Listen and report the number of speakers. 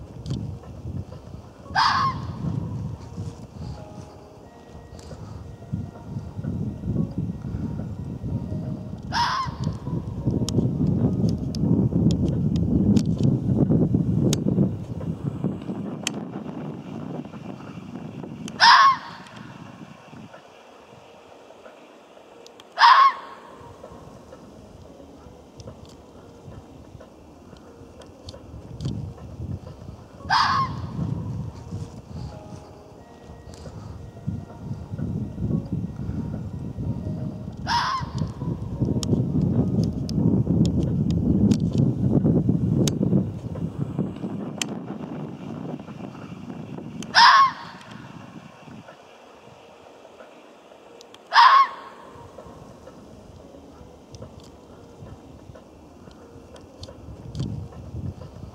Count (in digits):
0